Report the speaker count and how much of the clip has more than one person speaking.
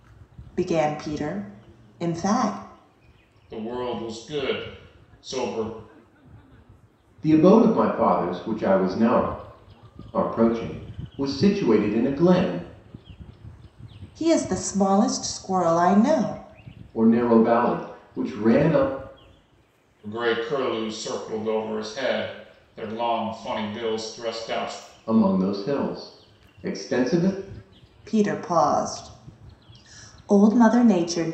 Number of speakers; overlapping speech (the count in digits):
3, no overlap